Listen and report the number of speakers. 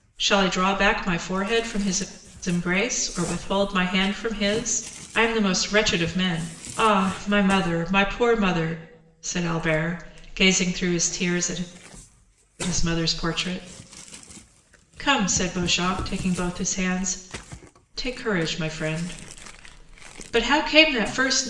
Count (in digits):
1